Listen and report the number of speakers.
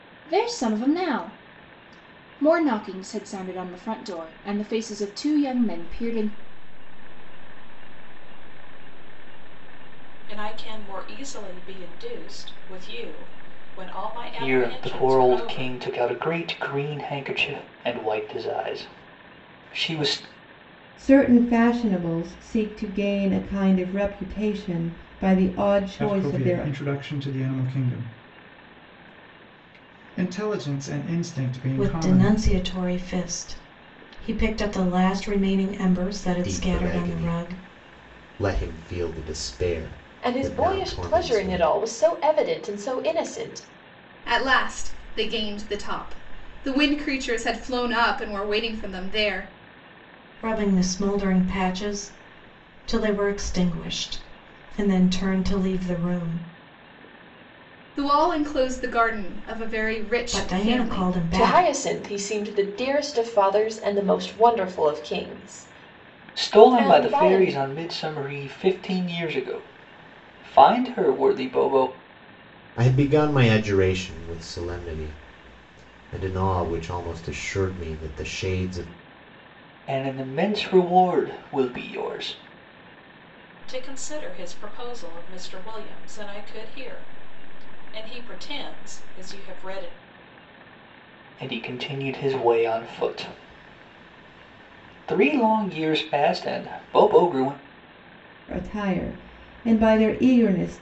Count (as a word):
ten